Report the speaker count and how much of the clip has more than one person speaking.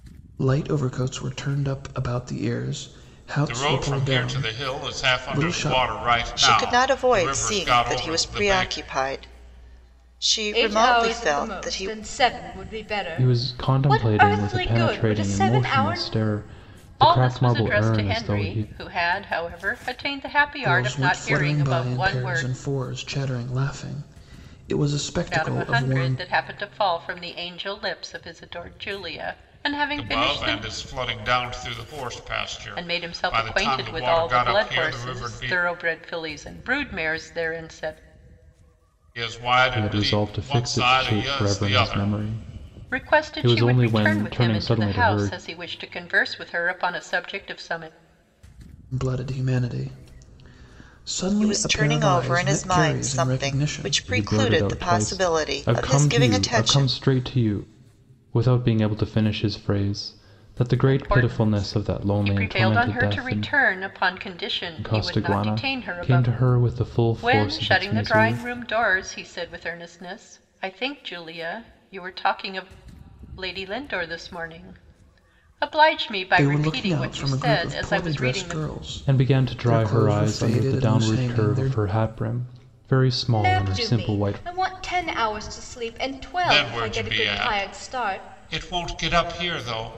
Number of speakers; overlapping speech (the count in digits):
6, about 46%